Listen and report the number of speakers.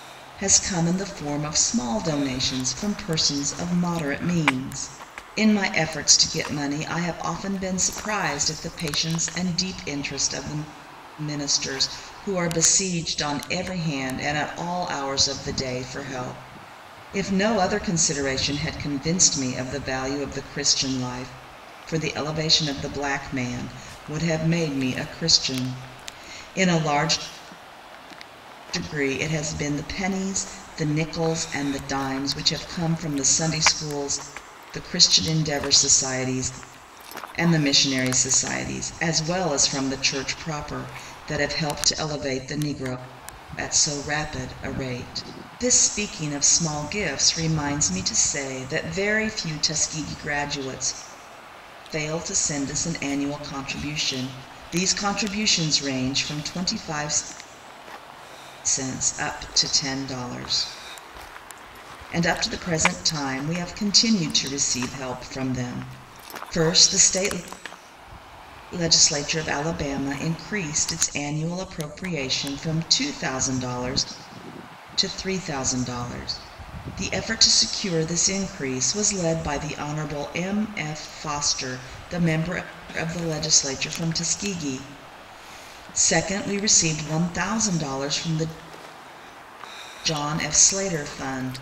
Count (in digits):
1